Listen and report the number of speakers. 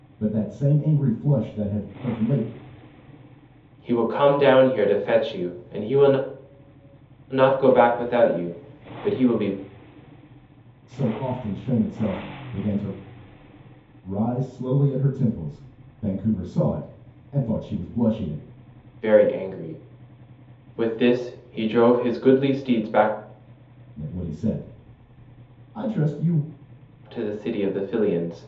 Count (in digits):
2